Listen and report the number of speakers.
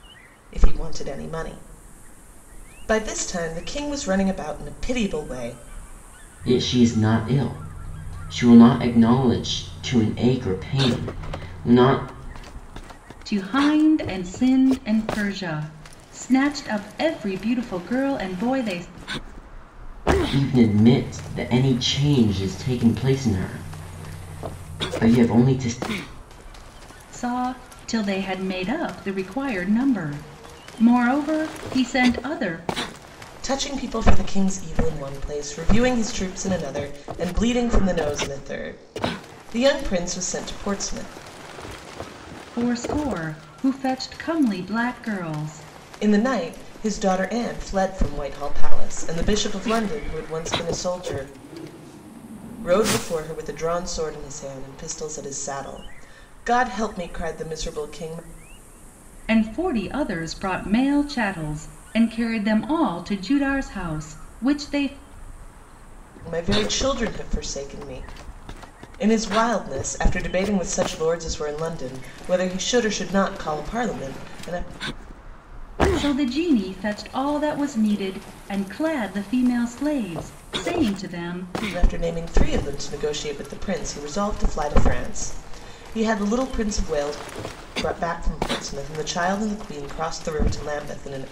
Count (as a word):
three